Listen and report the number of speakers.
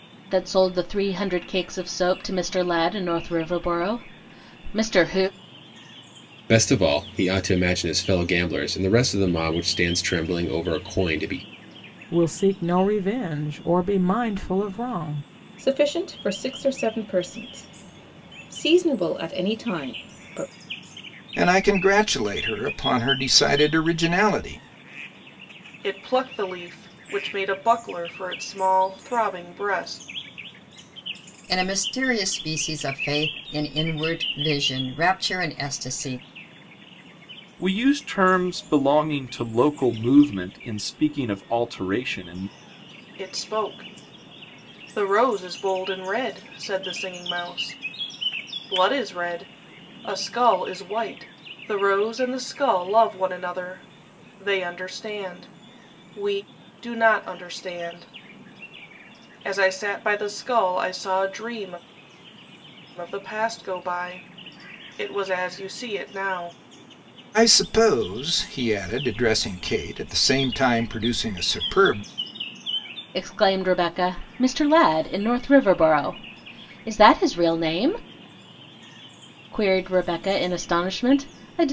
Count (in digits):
8